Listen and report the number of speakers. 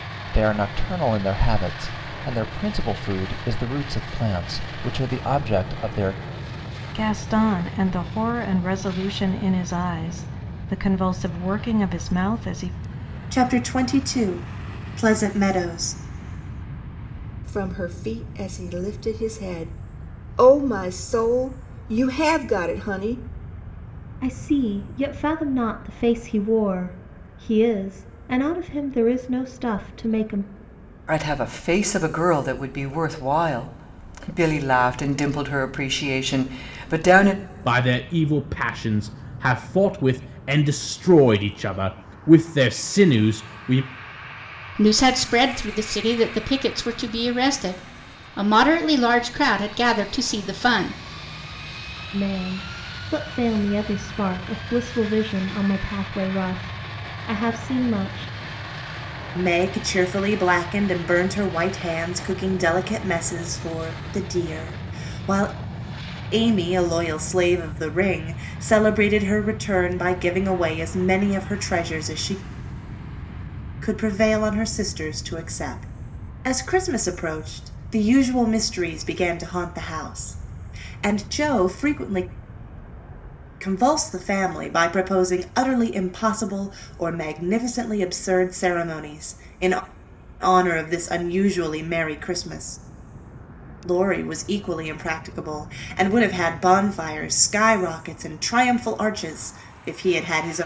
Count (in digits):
8